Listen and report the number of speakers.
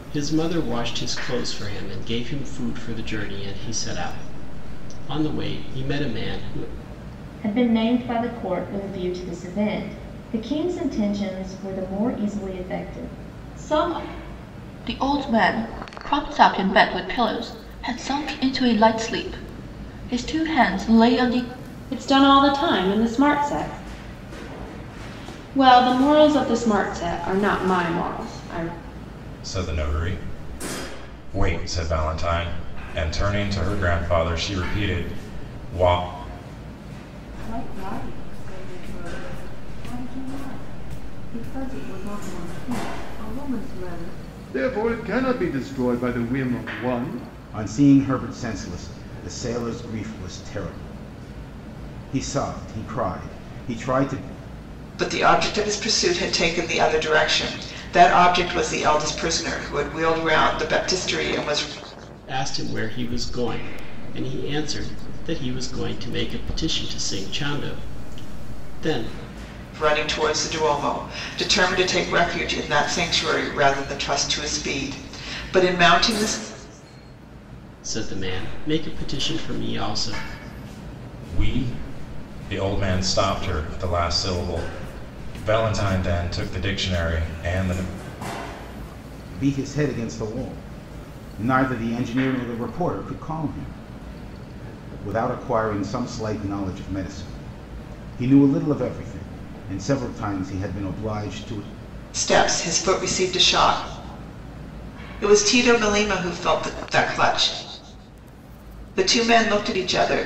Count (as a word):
nine